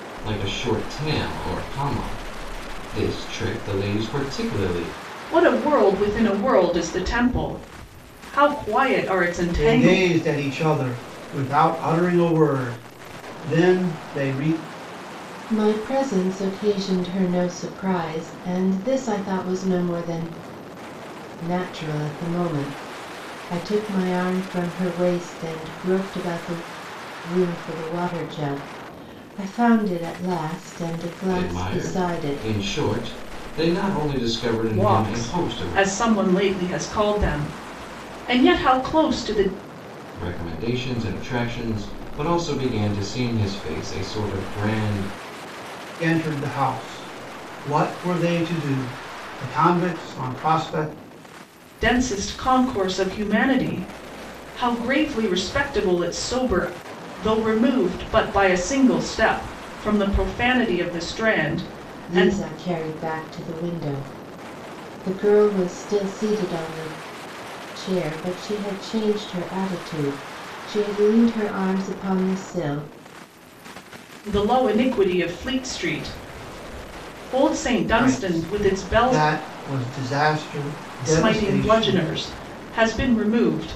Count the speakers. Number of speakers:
4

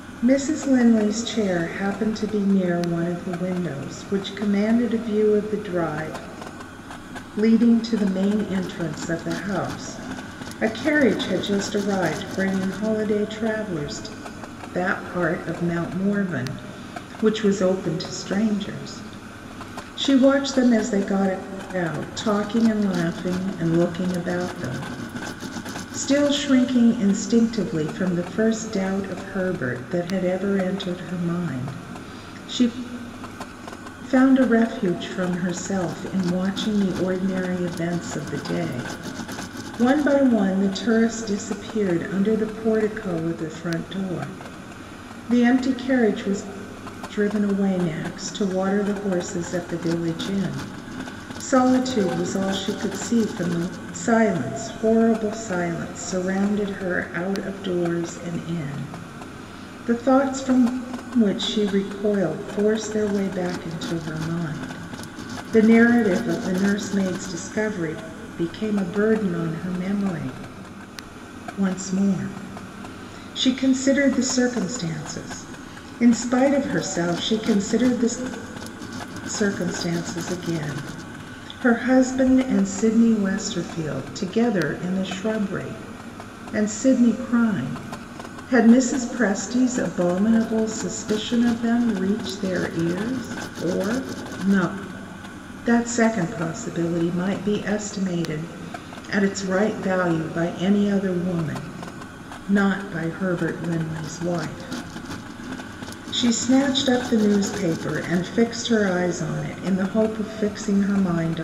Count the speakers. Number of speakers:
1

